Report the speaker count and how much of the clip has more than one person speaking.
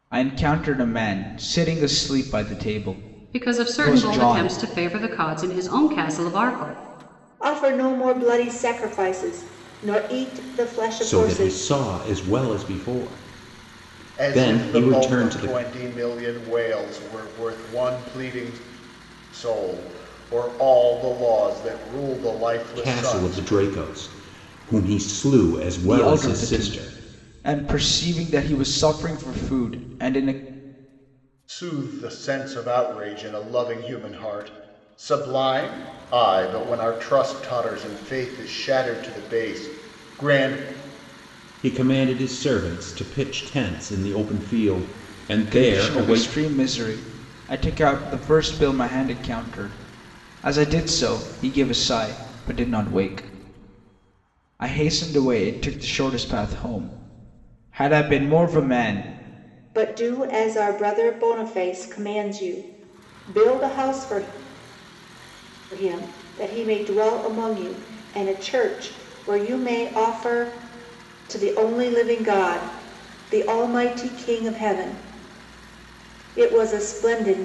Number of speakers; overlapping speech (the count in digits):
5, about 8%